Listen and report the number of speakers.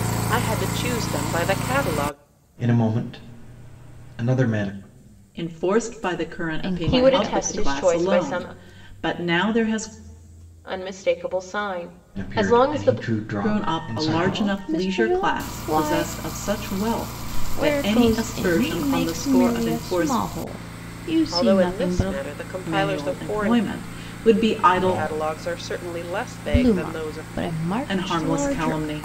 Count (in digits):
5